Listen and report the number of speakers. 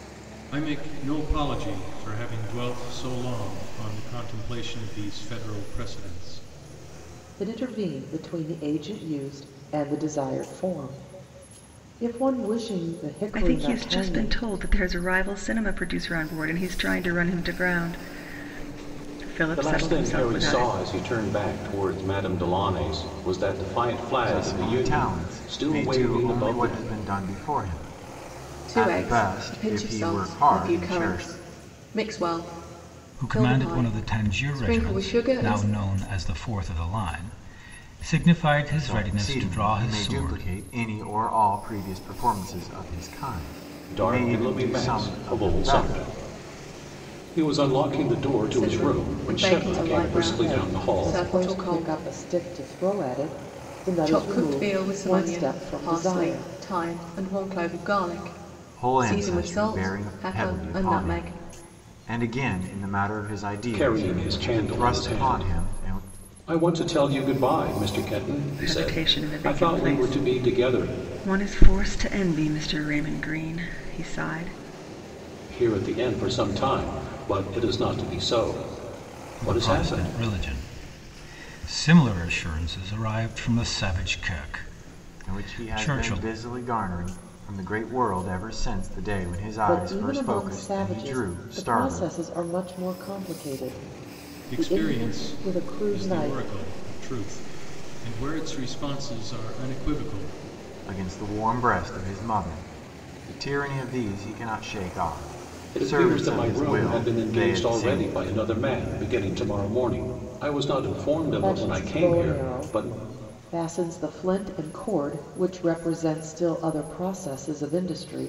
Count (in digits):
7